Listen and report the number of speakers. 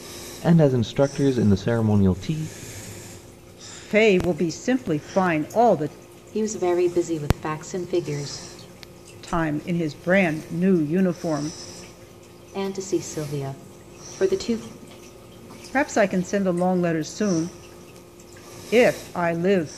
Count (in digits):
3